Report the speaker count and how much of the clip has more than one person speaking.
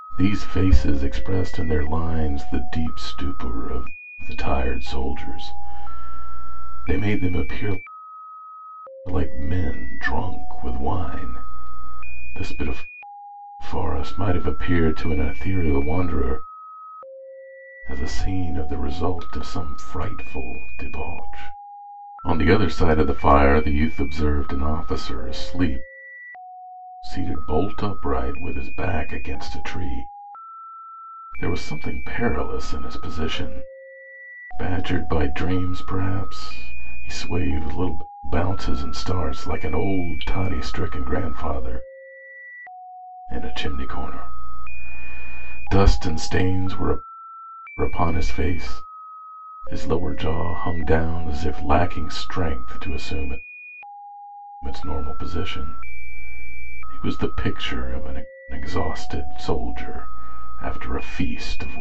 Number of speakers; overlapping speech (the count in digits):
1, no overlap